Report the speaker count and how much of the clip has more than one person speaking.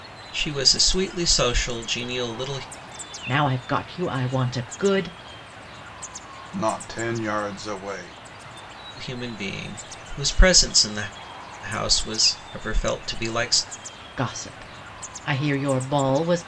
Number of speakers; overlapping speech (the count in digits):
3, no overlap